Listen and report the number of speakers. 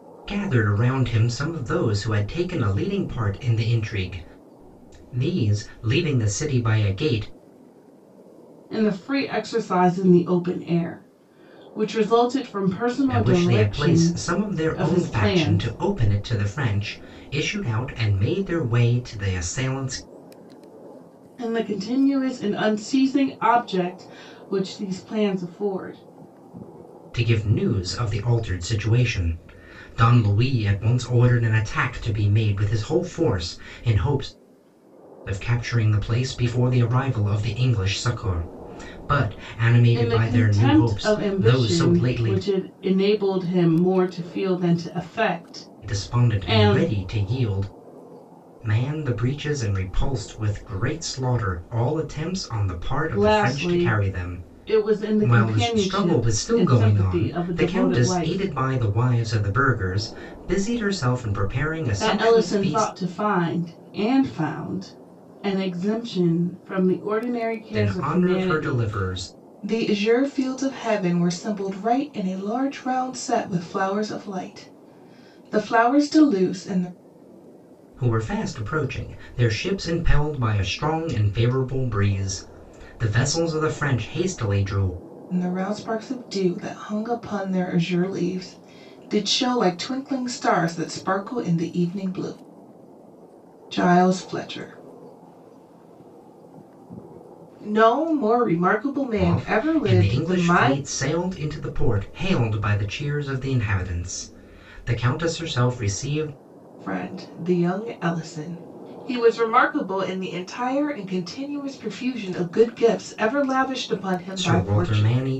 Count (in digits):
2